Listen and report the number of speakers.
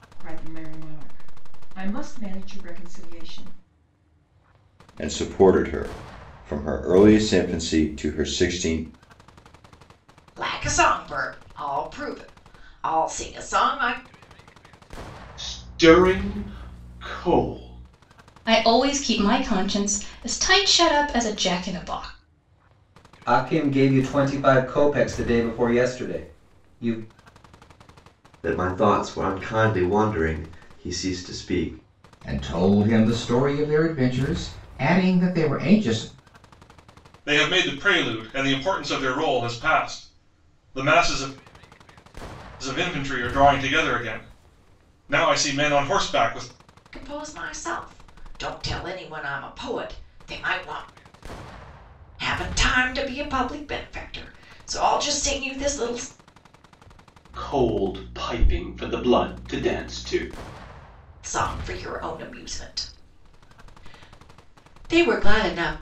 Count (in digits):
9